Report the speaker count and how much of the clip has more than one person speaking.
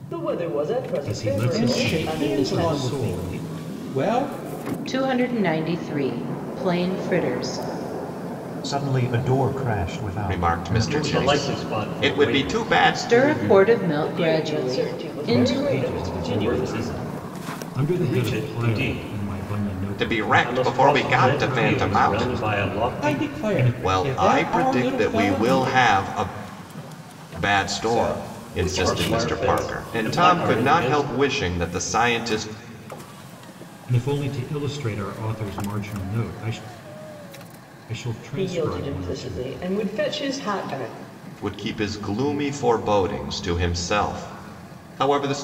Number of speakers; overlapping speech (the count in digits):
7, about 46%